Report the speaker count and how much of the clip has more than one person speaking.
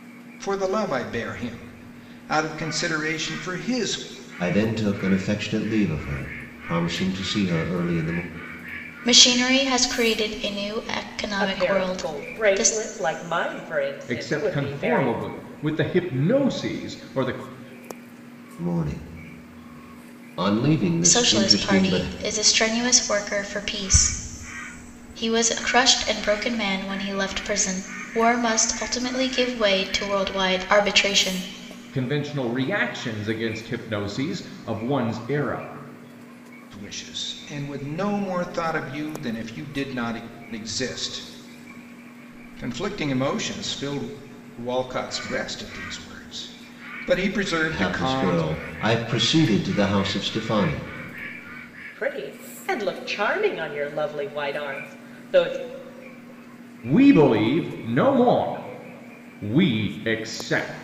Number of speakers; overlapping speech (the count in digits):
5, about 7%